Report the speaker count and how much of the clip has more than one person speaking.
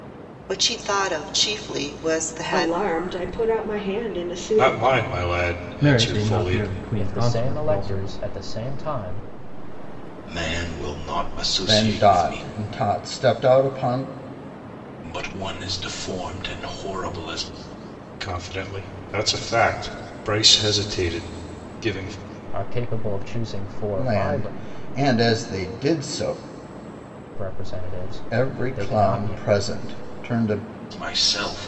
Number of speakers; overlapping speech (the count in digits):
7, about 17%